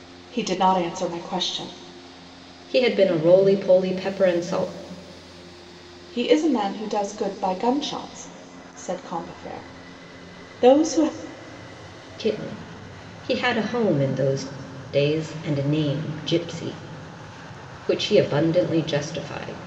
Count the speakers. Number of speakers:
2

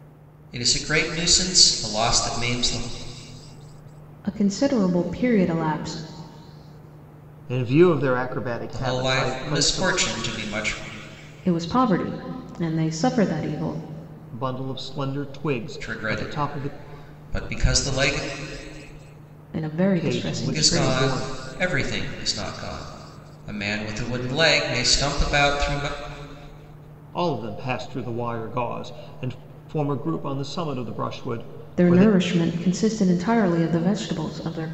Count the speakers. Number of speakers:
3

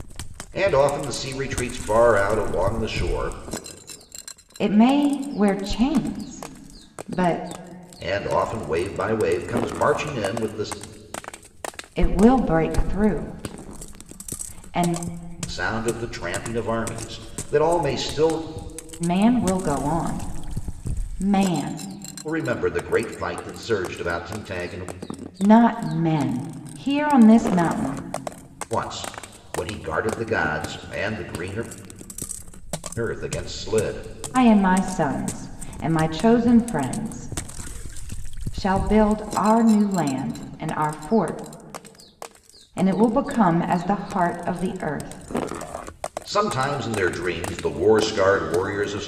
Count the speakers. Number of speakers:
2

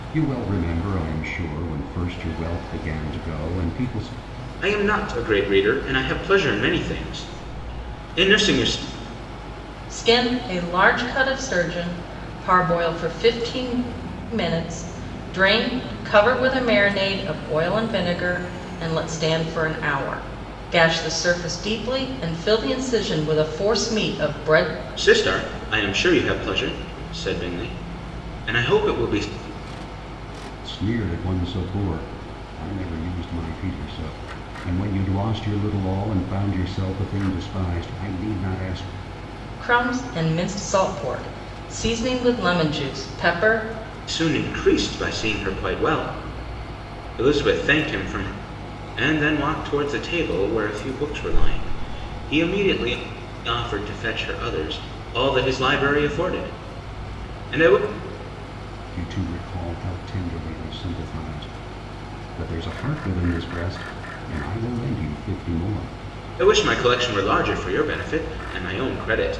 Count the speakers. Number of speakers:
3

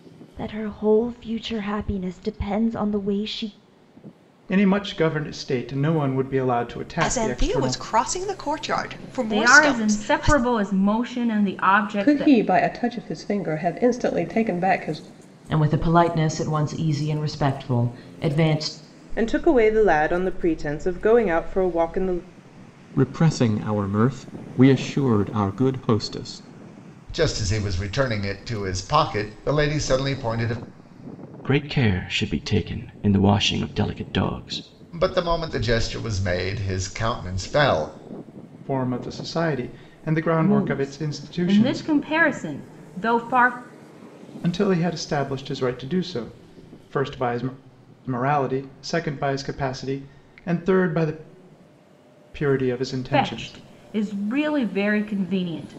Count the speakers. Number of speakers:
10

